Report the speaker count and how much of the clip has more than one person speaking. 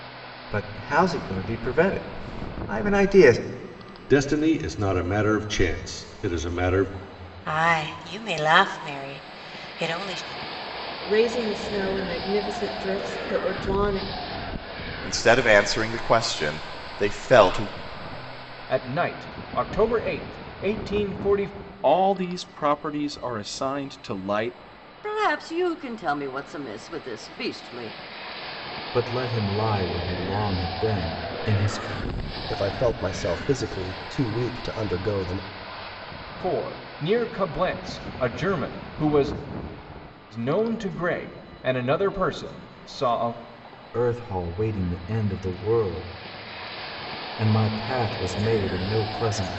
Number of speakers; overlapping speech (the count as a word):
ten, no overlap